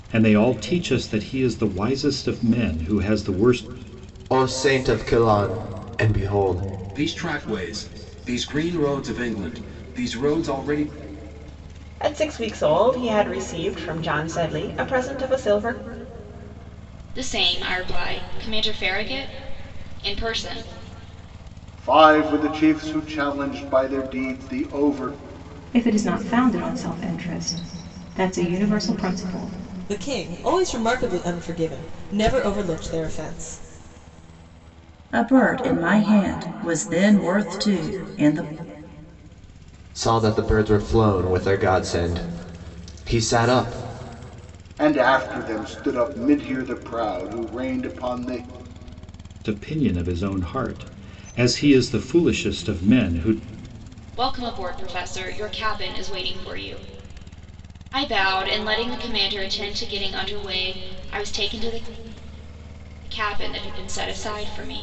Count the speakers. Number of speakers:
9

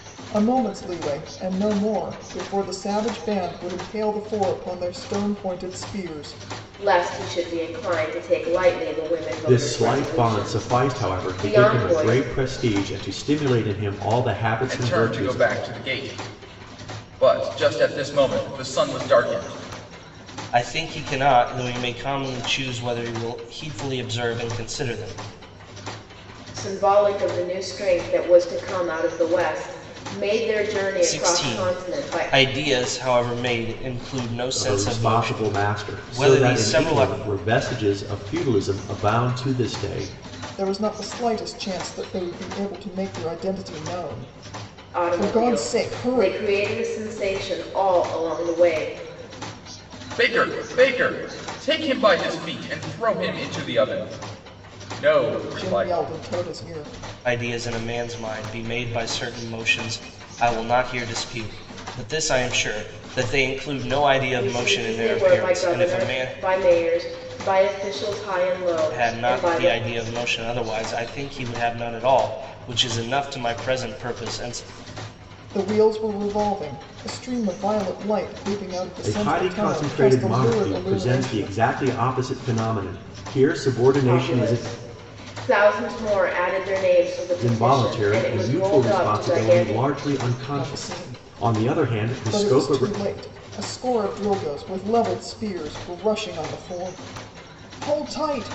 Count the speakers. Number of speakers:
5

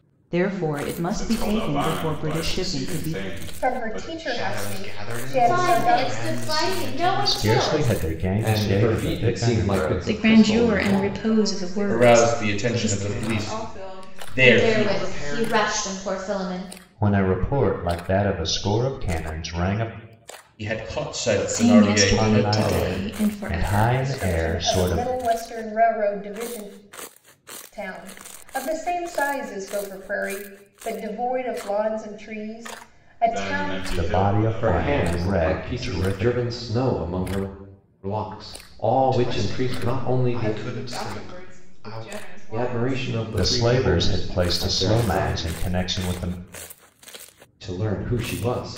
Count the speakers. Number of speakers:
10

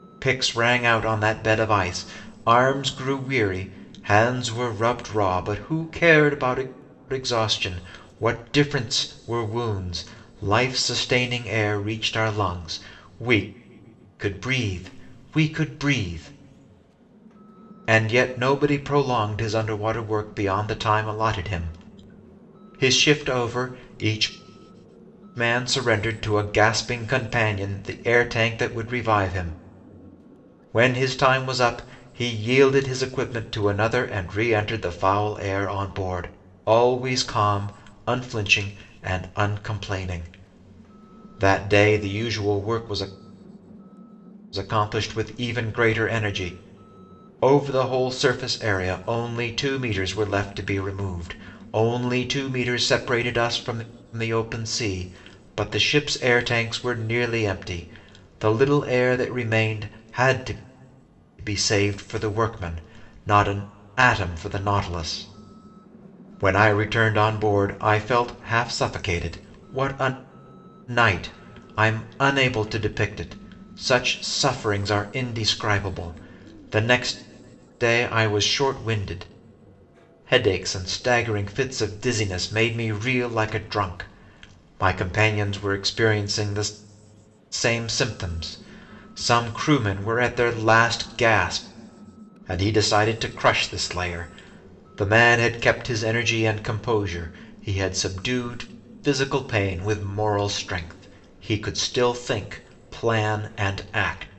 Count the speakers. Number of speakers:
1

